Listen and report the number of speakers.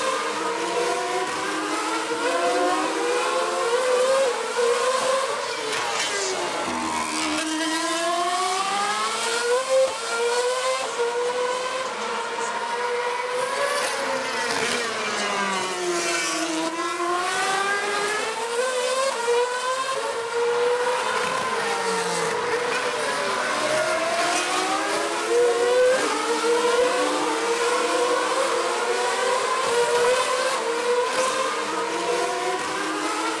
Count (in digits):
0